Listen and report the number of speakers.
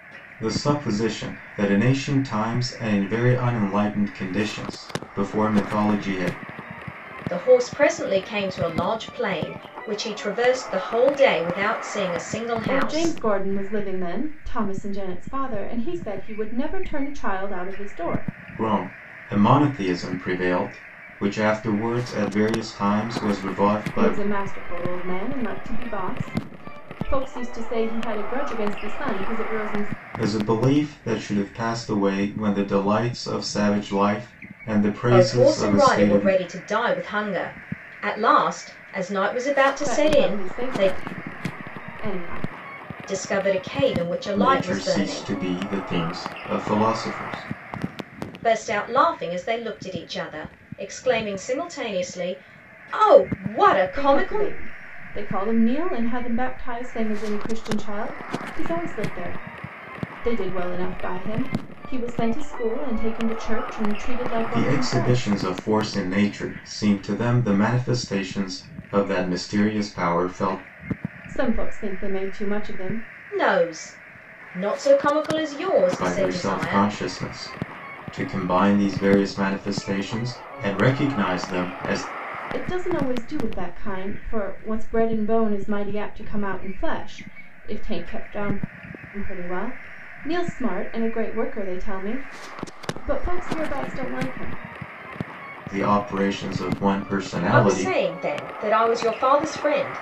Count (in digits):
3